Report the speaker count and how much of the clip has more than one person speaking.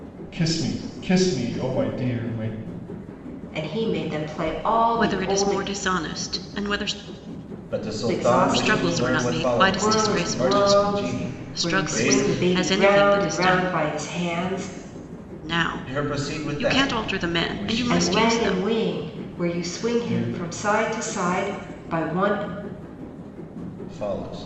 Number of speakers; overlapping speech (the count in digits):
4, about 39%